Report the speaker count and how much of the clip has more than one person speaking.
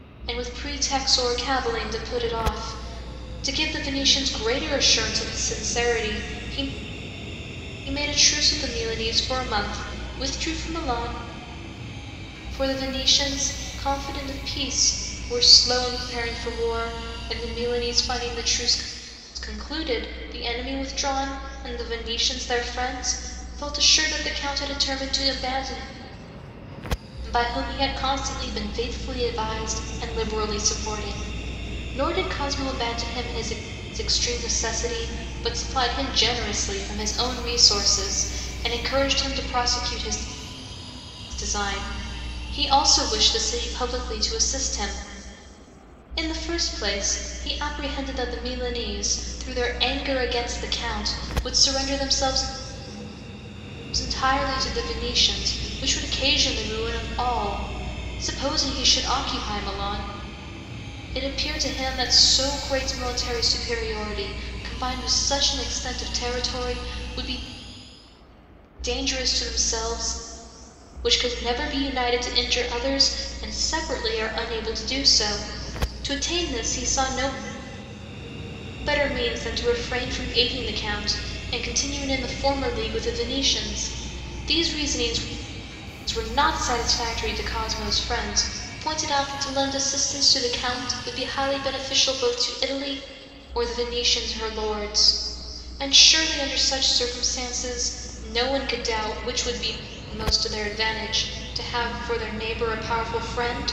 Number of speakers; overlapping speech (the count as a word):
one, no overlap